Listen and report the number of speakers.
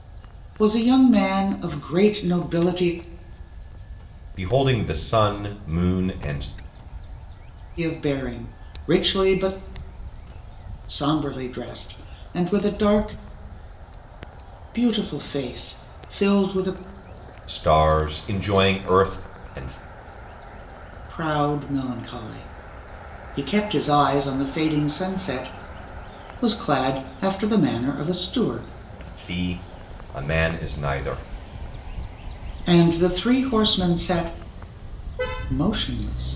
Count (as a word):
two